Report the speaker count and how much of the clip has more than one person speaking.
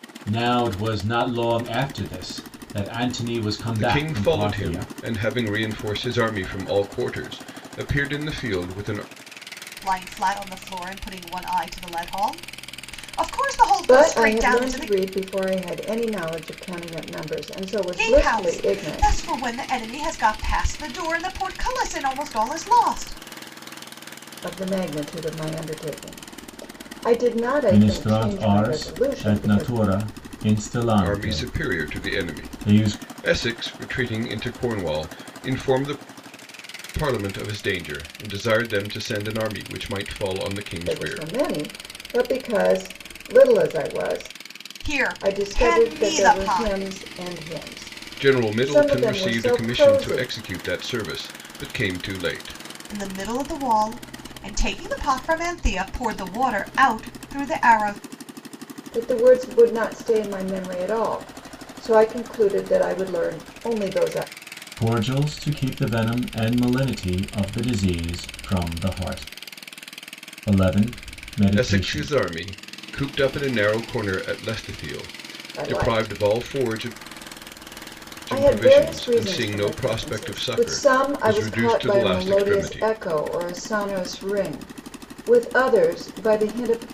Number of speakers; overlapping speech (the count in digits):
4, about 22%